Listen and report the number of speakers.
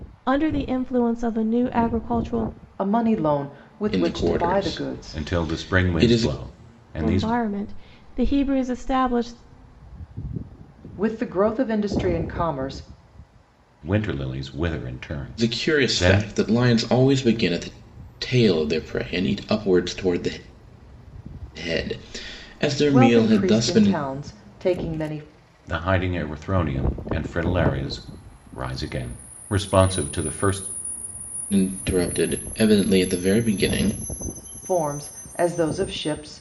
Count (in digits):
4